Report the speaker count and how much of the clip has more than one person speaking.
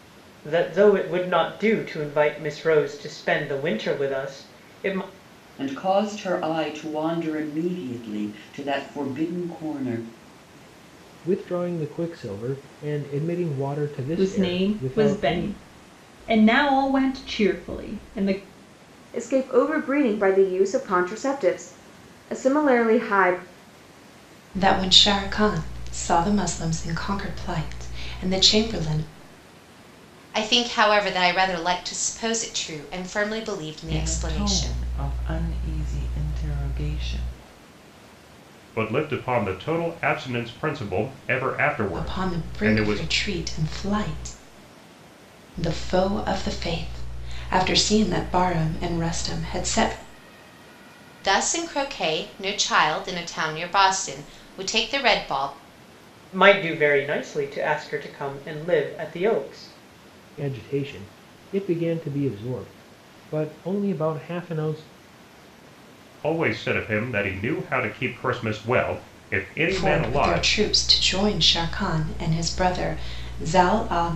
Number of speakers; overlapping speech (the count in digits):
9, about 6%